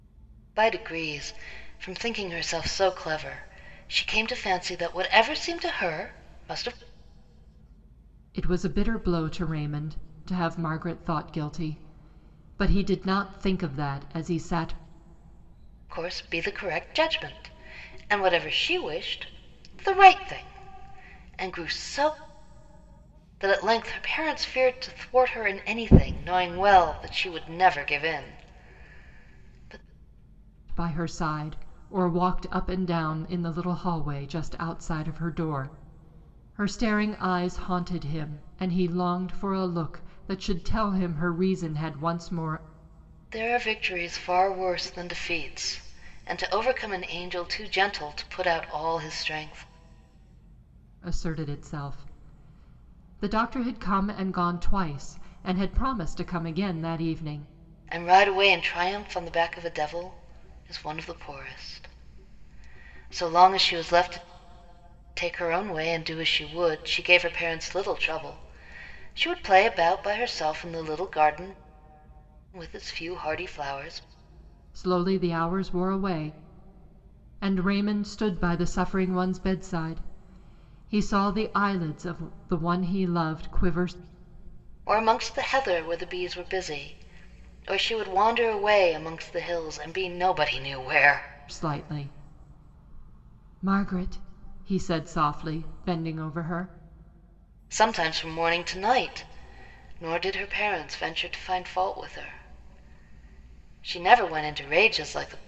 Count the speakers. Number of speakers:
two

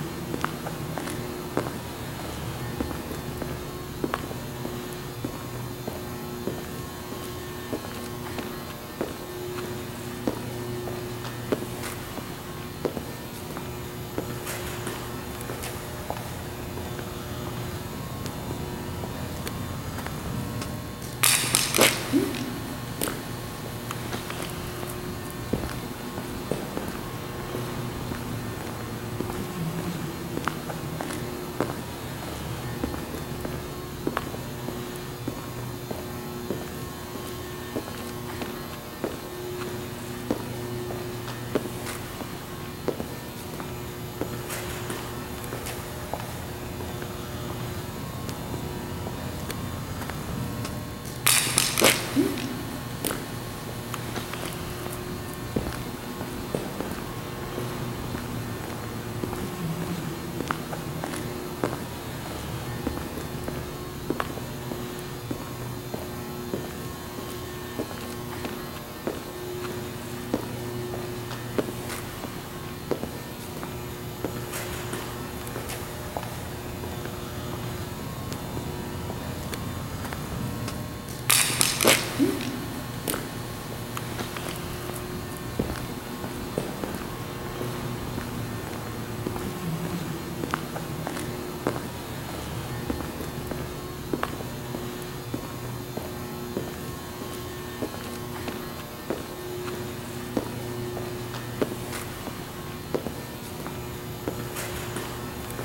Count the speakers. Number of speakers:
zero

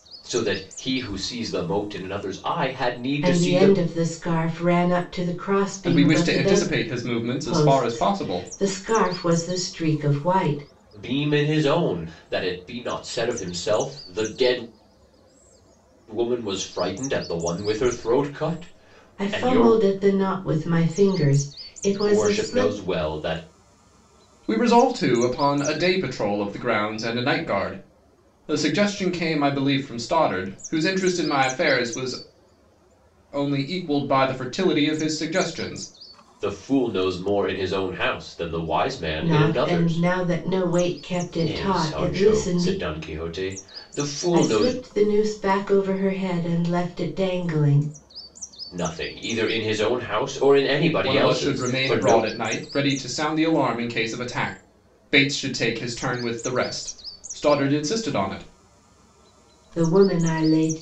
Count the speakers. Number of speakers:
three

